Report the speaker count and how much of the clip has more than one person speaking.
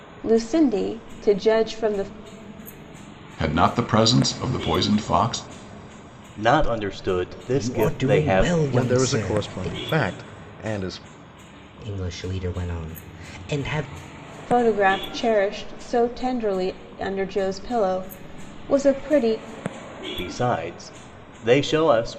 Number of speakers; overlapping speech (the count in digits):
5, about 10%